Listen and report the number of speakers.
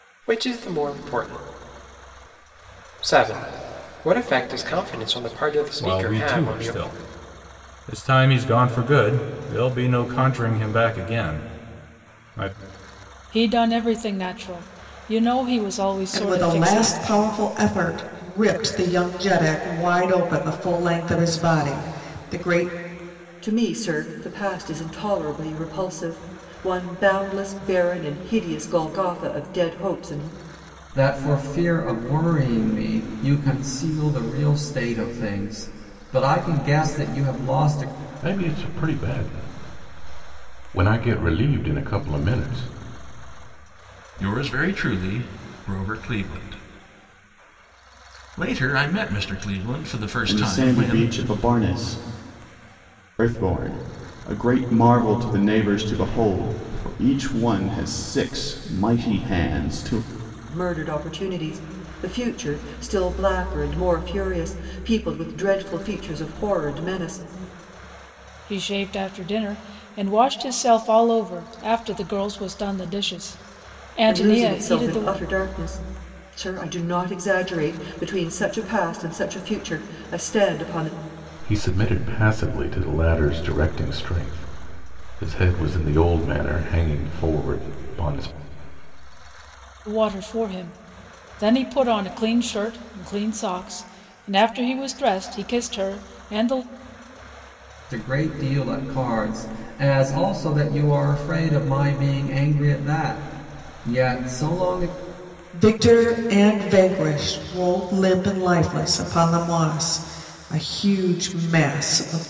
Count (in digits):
9